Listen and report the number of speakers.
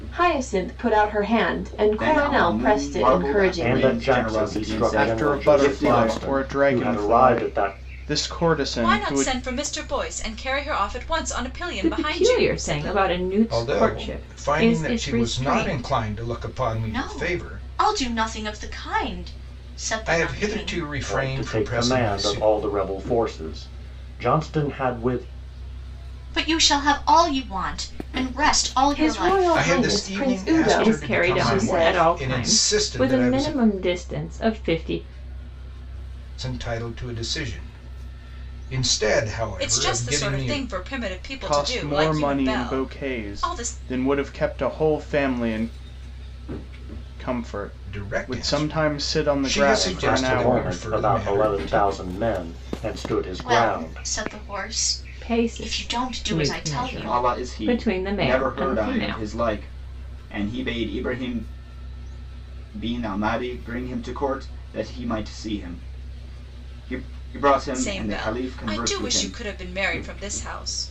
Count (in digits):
8